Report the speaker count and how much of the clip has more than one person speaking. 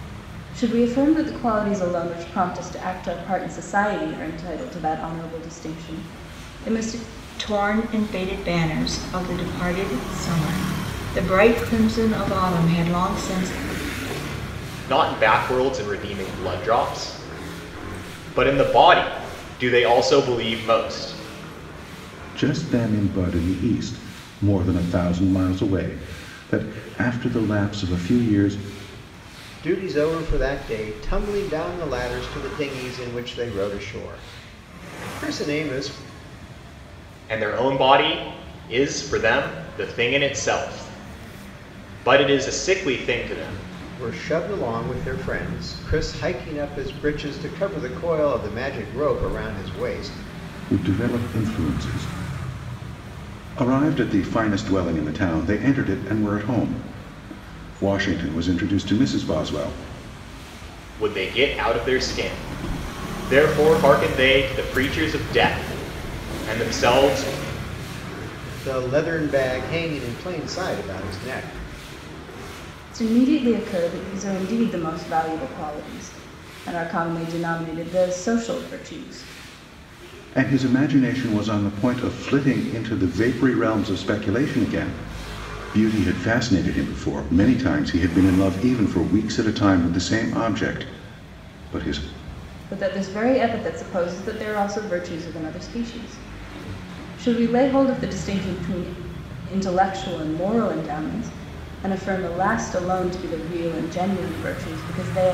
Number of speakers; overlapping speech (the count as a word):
five, no overlap